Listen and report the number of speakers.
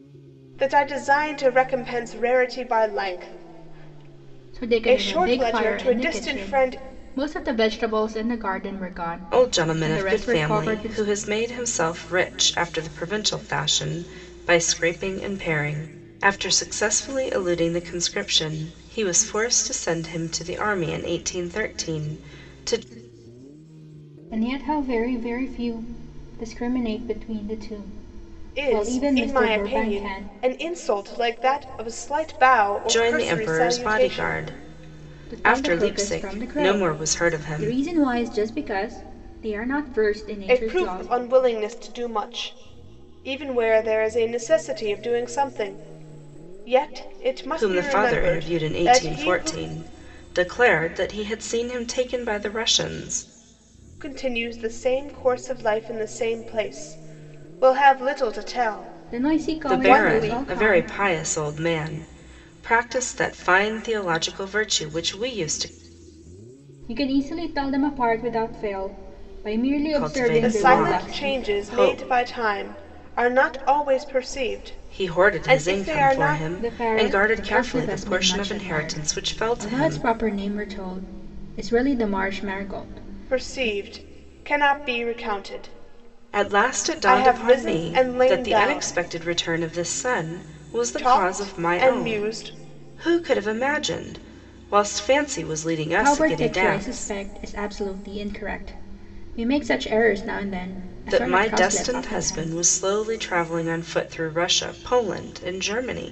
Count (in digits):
3